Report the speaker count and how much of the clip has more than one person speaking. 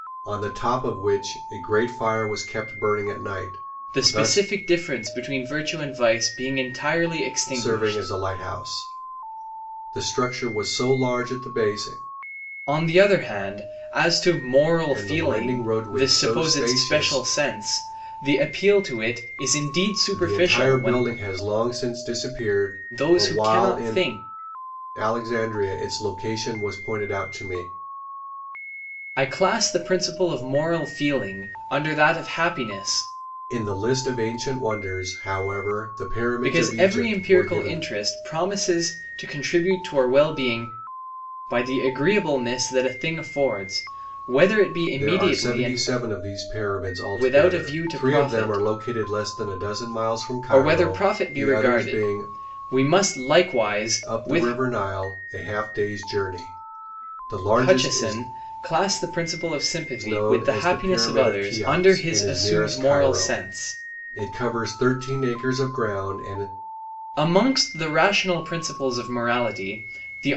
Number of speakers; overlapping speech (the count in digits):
2, about 23%